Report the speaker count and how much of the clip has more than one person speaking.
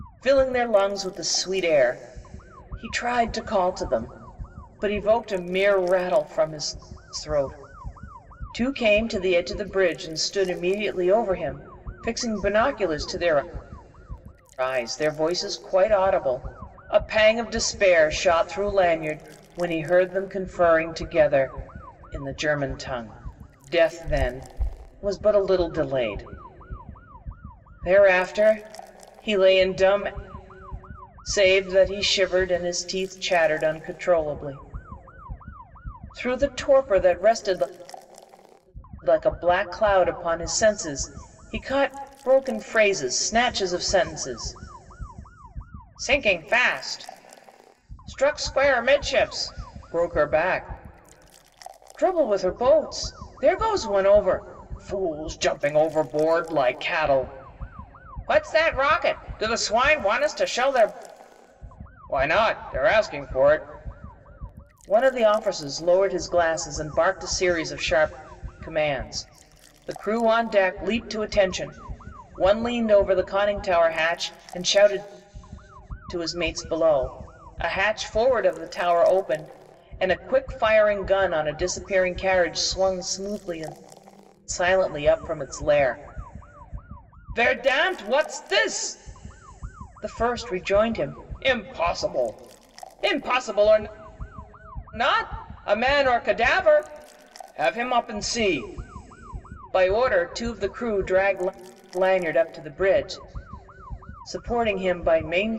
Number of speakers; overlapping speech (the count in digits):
1, no overlap